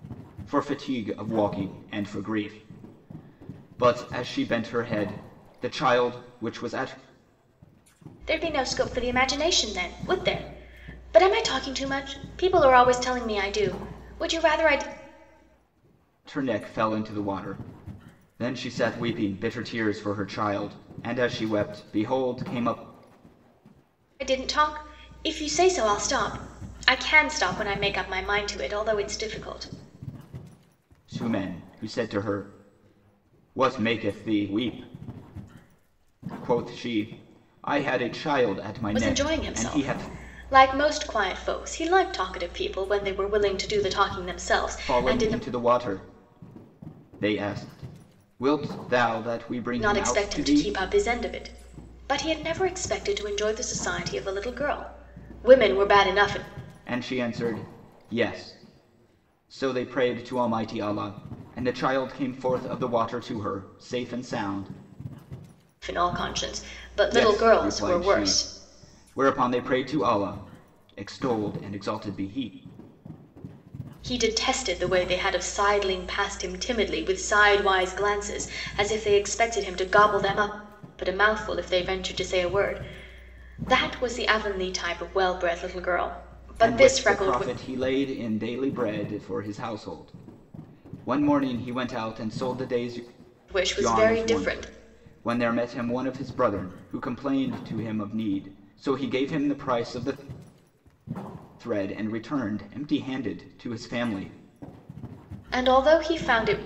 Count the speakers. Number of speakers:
2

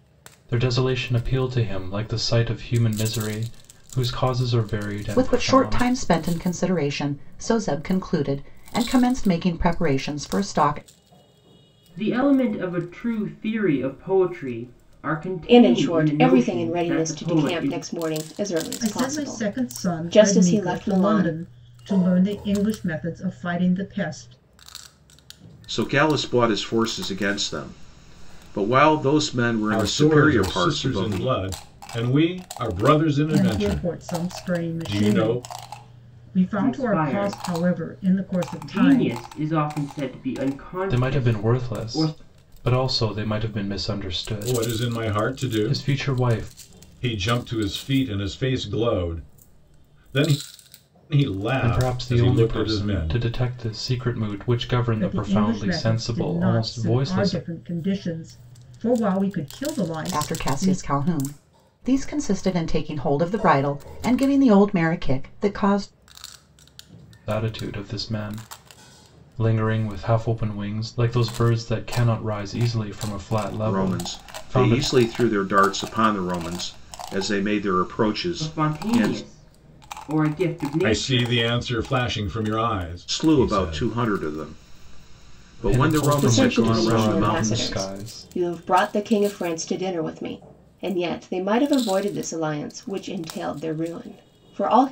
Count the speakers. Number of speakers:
7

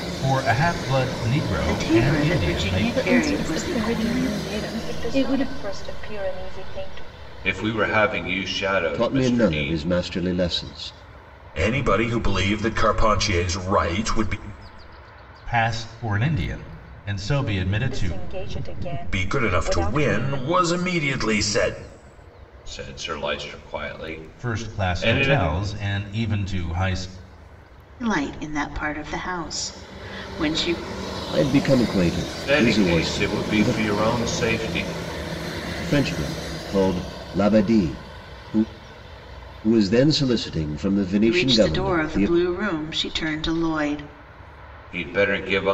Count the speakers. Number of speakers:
7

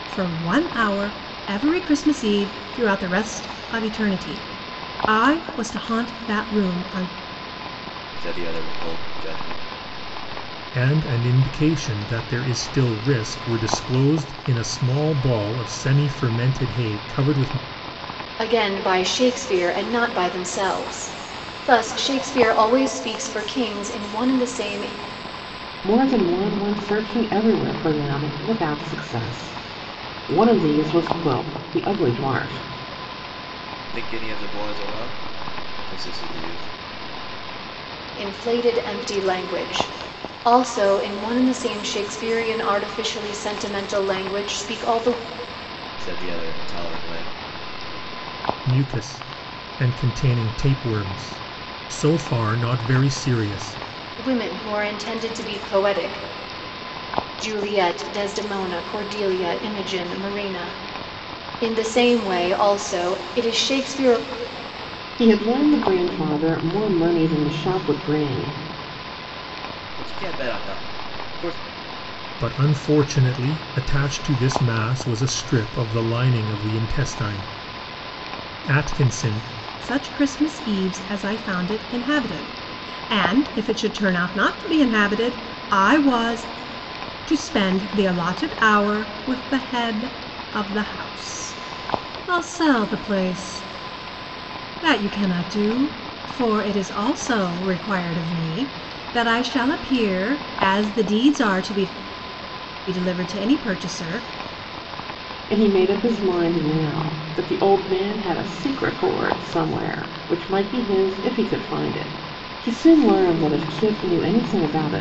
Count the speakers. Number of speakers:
5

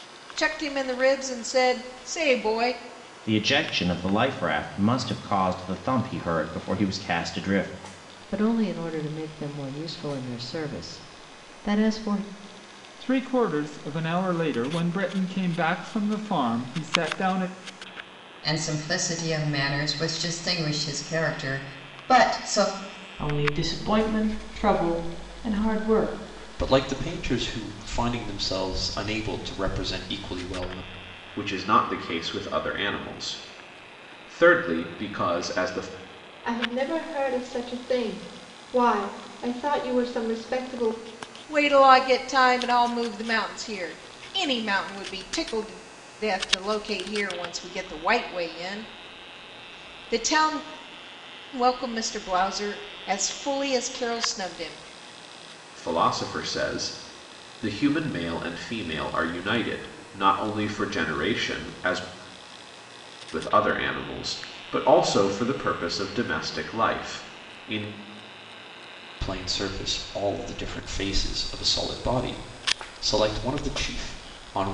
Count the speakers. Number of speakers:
9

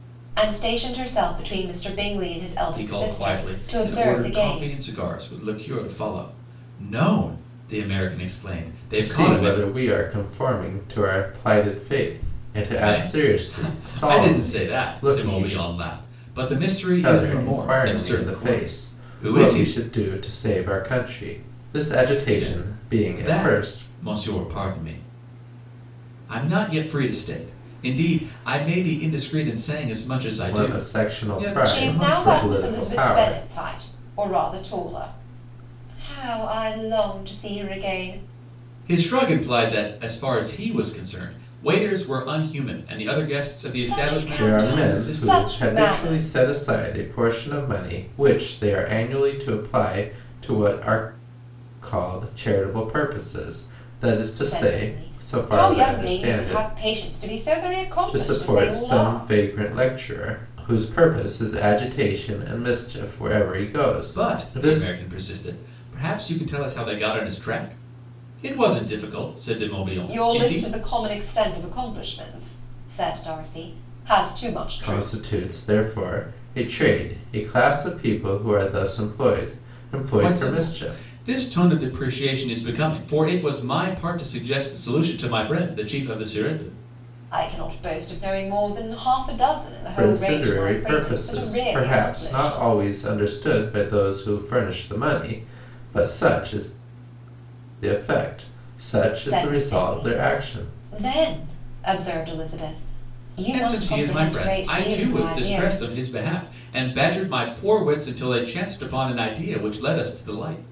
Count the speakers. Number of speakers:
3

